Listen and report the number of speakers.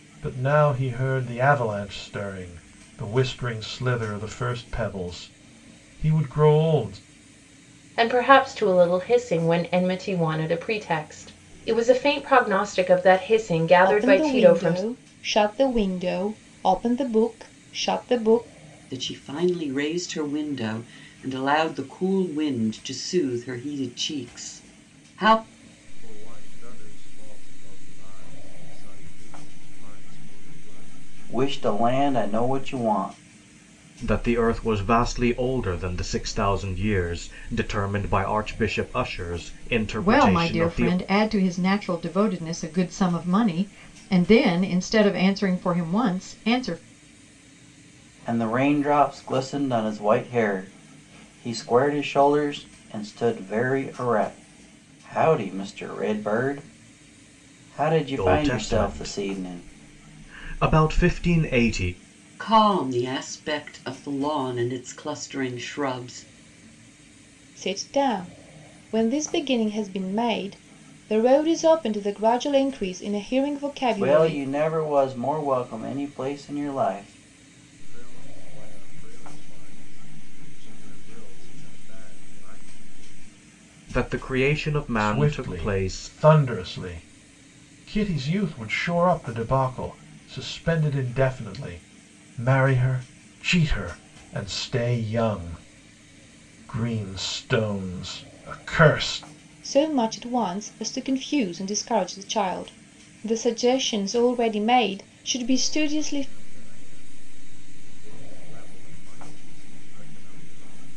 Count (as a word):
eight